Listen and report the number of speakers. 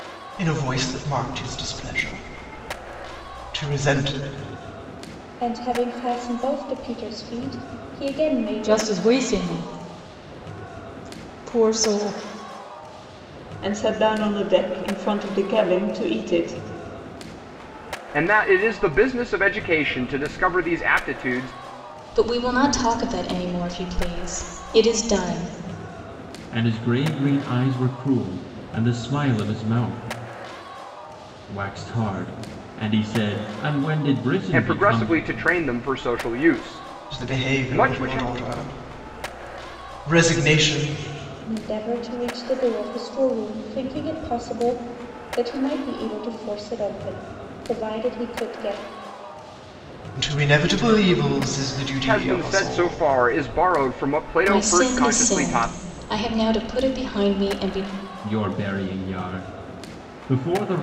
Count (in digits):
7